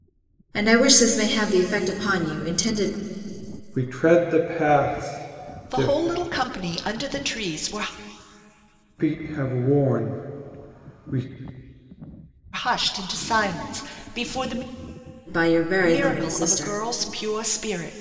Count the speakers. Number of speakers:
3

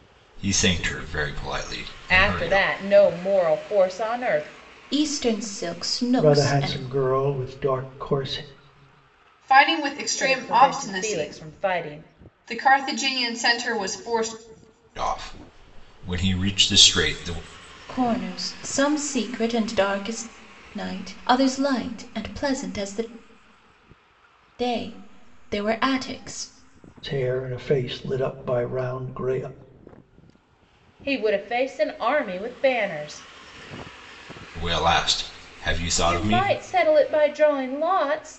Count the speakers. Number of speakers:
5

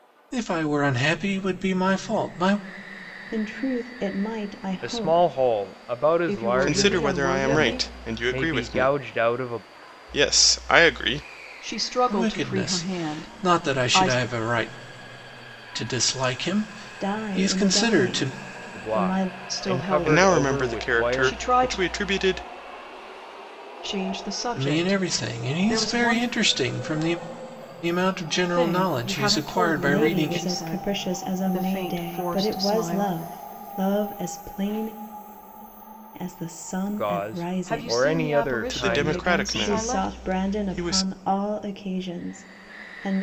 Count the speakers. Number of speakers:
5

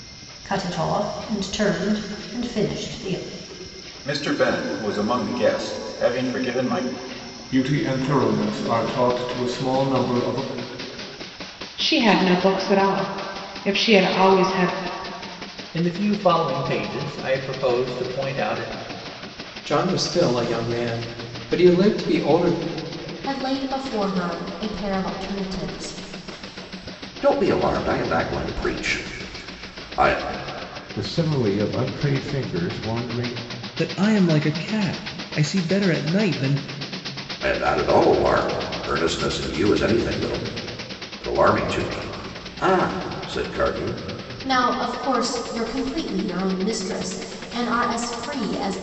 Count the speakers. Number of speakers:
10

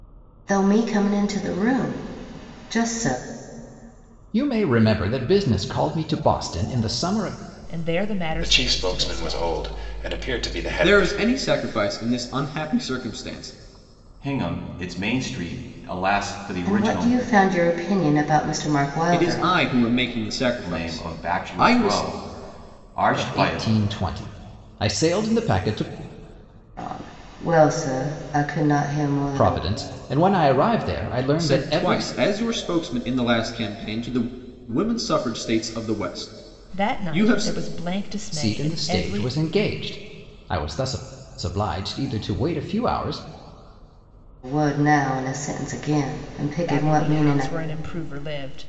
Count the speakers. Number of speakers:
6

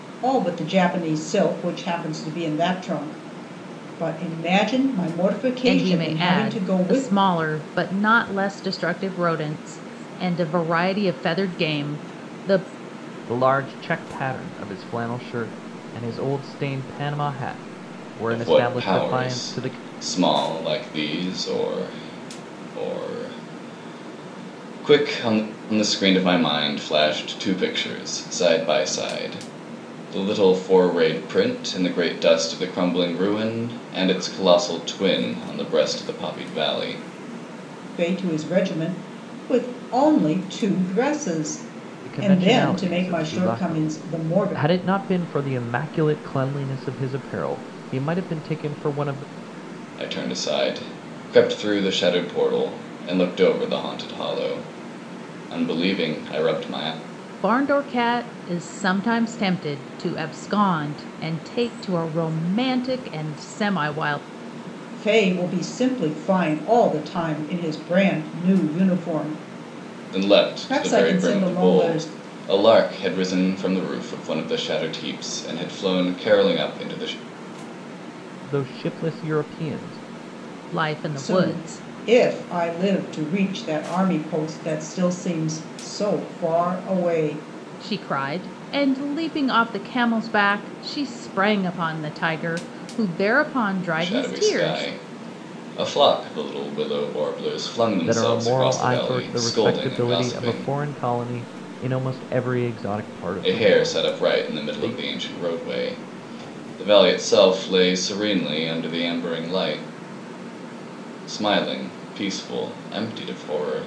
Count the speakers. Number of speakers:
4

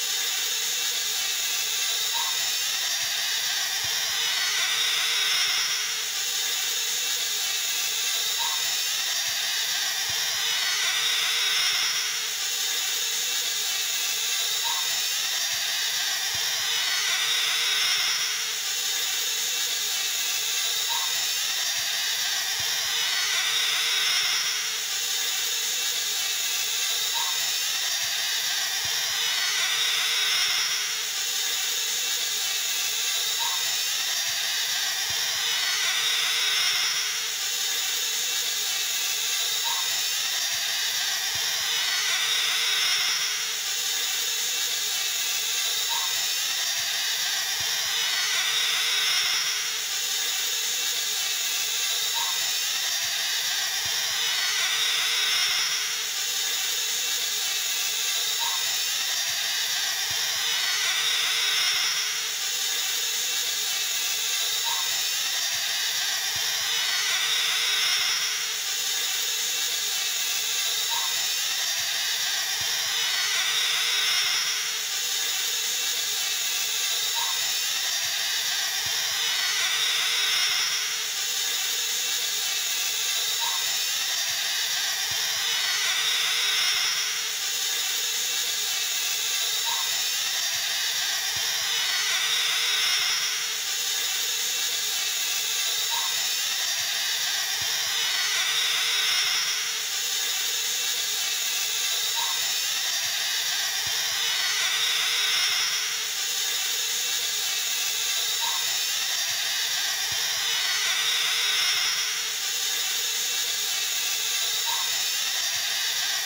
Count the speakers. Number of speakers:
0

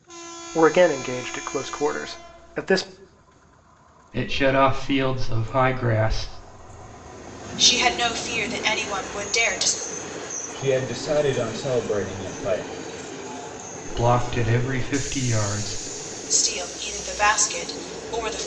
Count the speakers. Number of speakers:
4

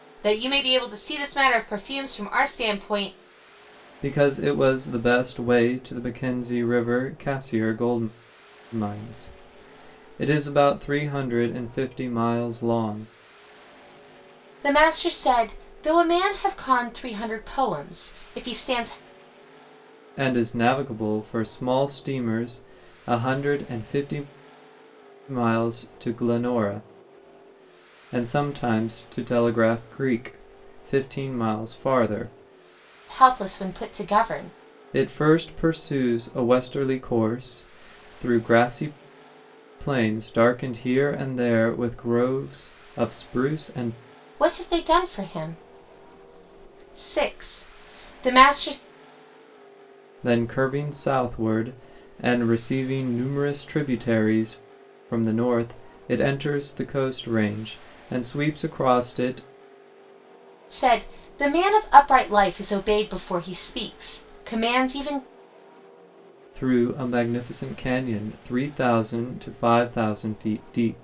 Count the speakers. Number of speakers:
2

